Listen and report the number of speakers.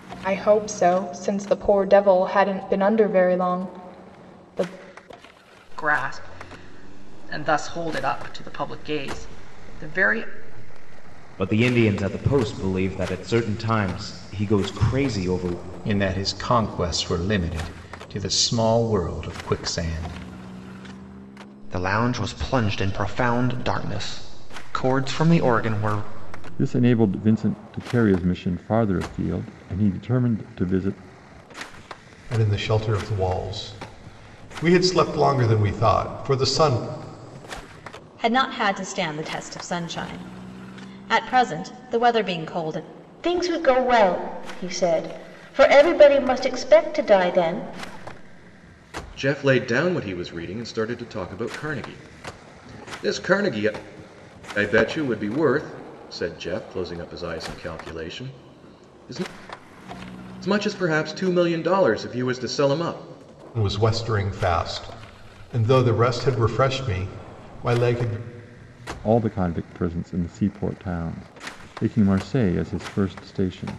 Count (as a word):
ten